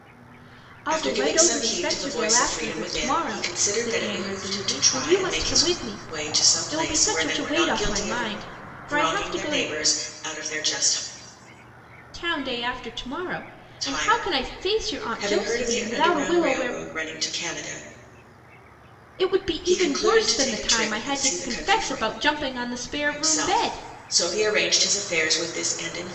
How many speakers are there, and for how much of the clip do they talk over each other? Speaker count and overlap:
two, about 54%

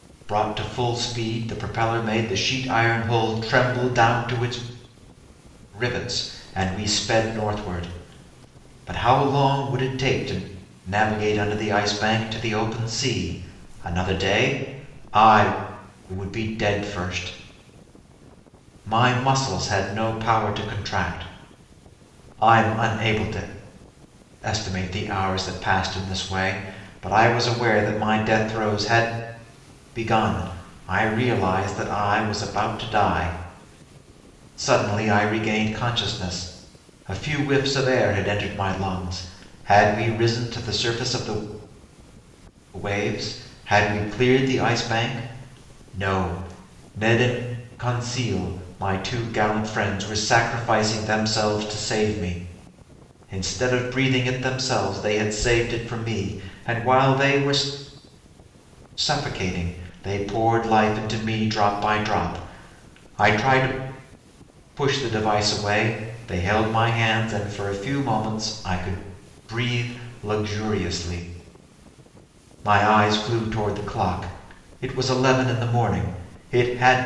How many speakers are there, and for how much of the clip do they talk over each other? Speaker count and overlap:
one, no overlap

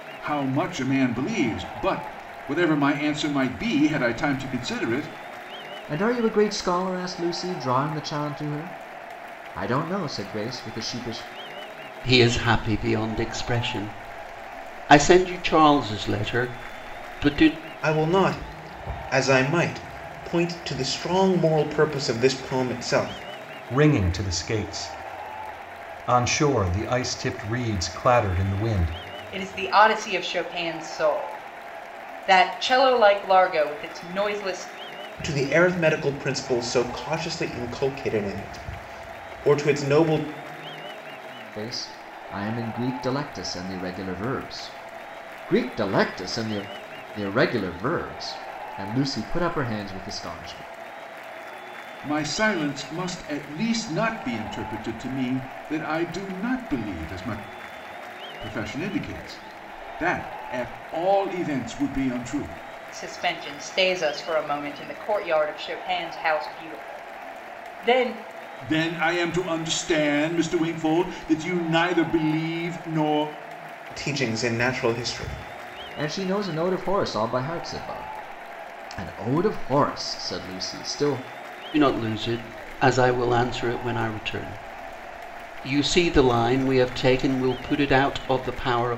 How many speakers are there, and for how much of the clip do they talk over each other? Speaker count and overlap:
six, no overlap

